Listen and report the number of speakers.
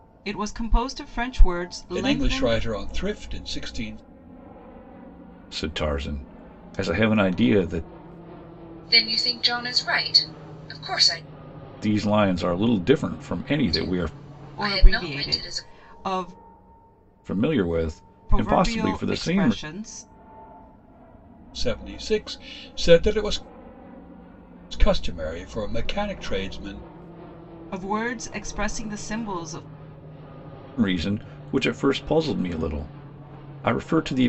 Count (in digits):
4